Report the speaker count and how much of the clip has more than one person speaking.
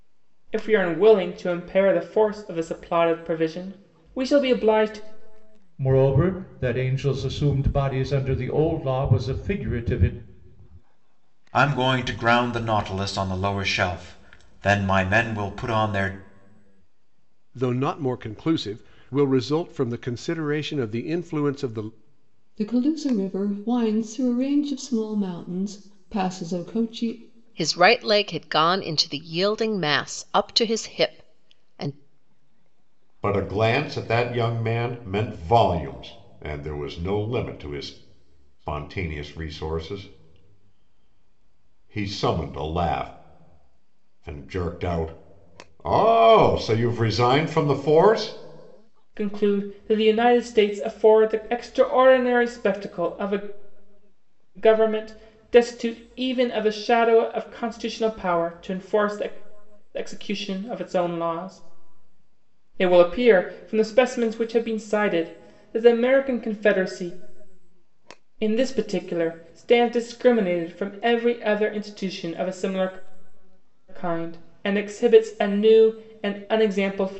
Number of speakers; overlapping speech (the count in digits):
7, no overlap